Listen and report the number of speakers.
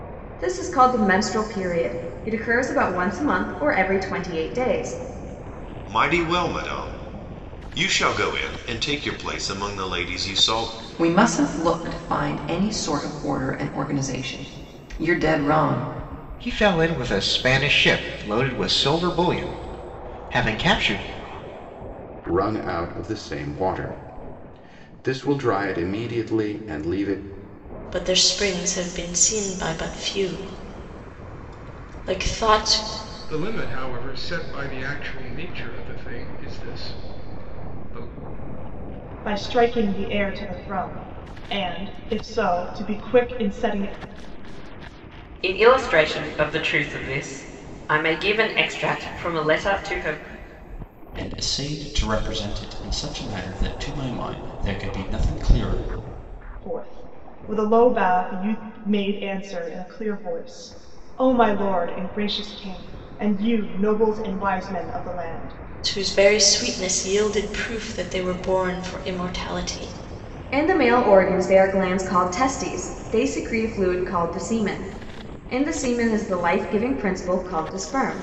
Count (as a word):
ten